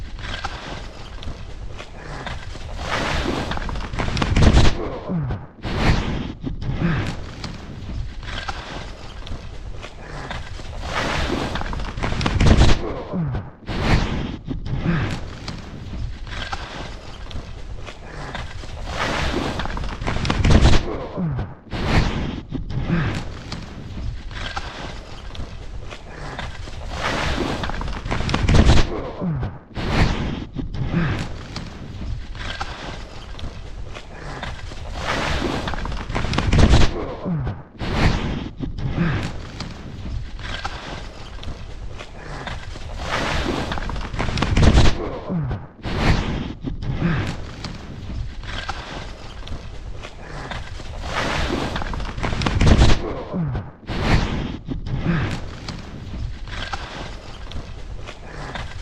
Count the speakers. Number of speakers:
zero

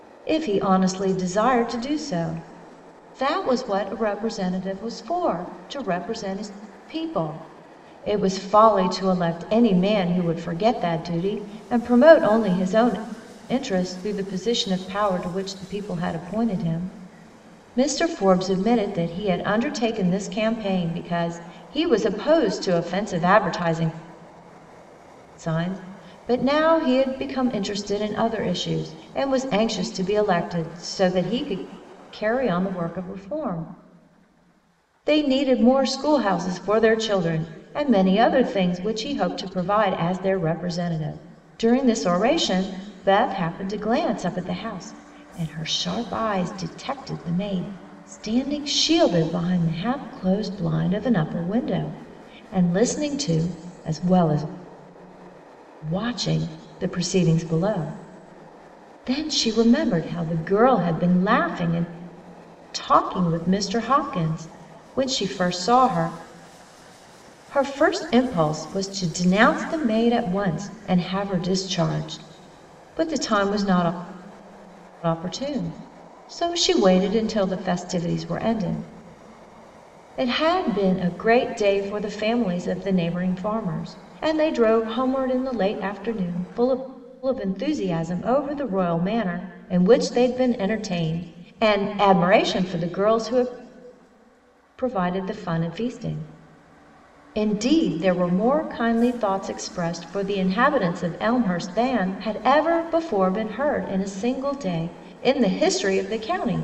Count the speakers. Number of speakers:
one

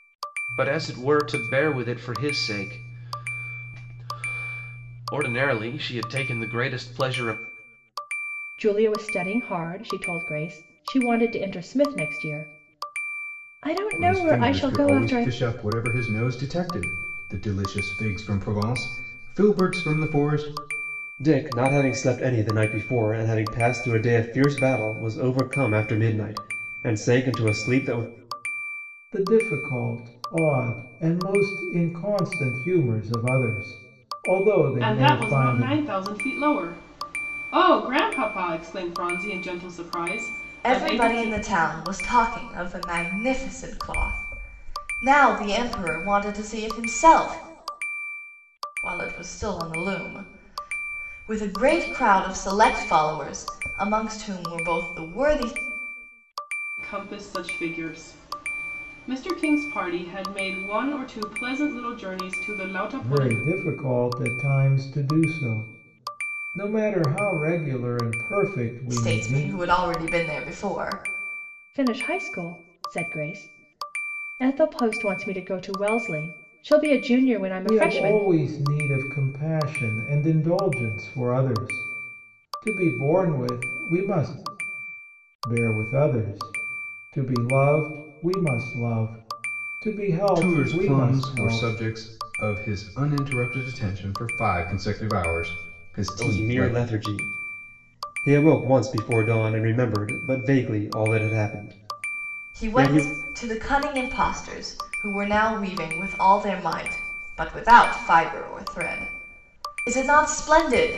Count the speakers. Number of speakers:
seven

